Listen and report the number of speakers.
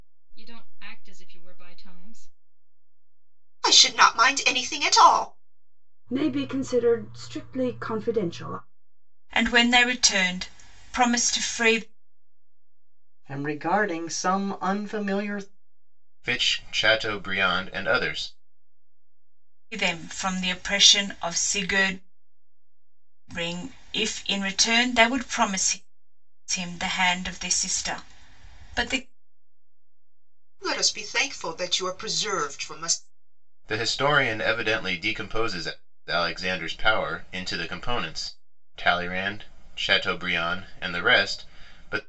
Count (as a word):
six